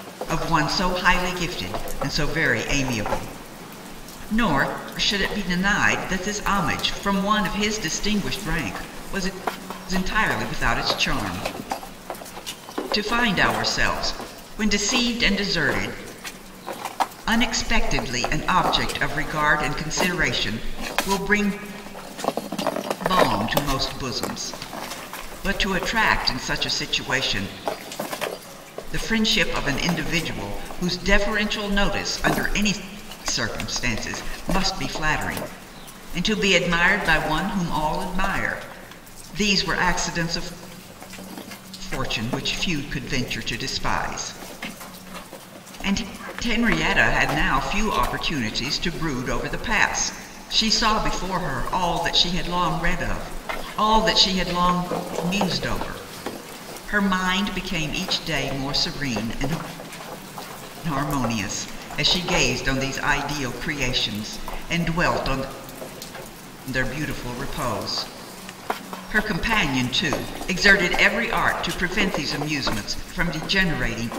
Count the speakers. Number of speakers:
1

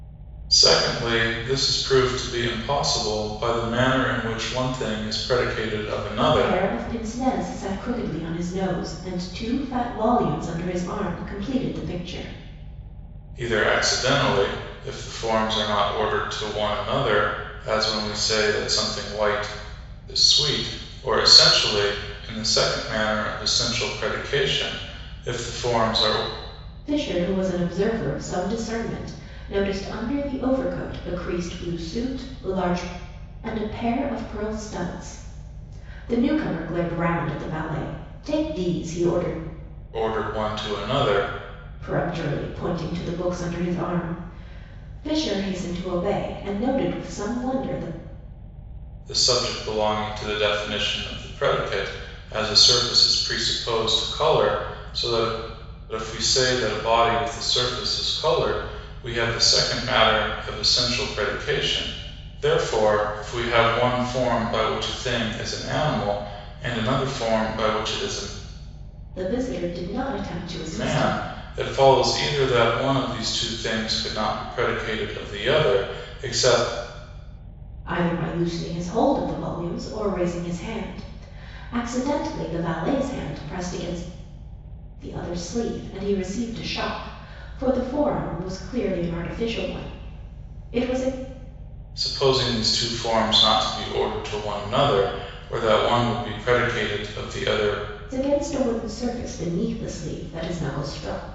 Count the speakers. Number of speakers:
2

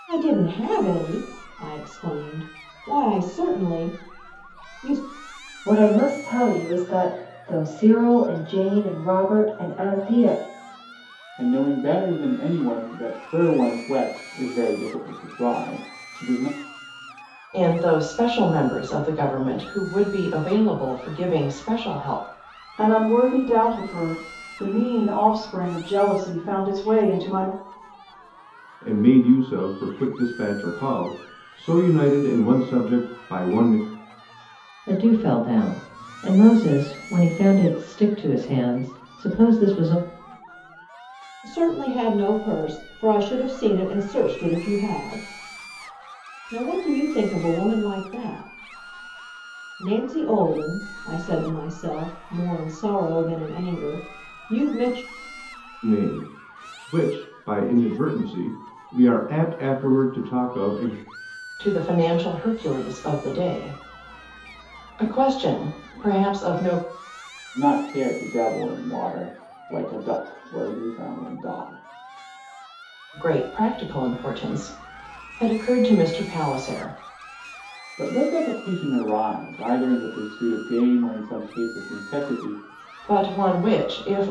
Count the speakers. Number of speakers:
7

